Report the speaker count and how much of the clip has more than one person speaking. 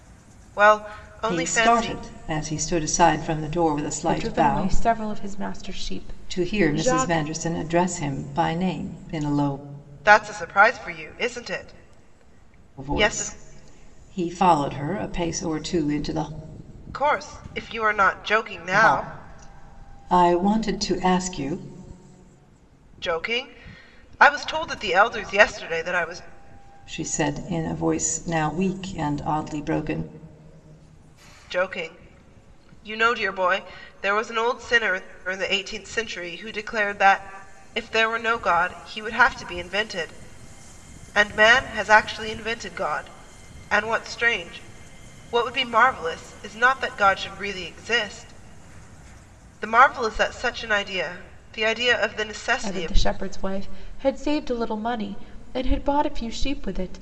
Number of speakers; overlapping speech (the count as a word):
three, about 7%